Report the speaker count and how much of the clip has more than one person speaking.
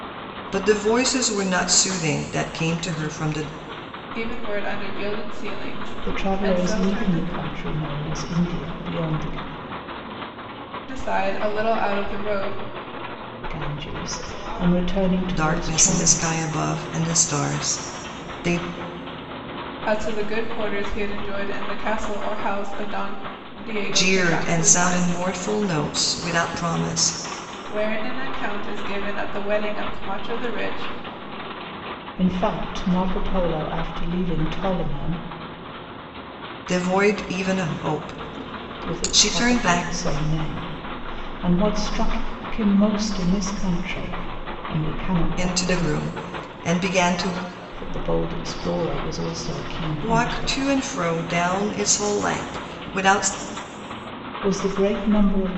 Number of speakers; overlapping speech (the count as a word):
three, about 11%